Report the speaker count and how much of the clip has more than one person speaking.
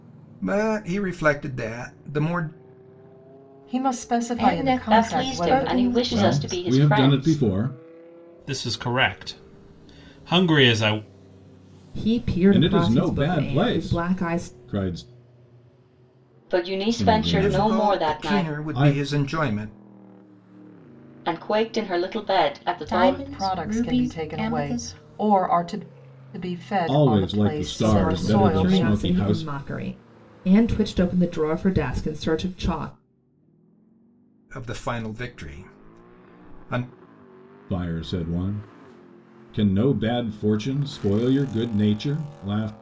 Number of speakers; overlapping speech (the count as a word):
seven, about 28%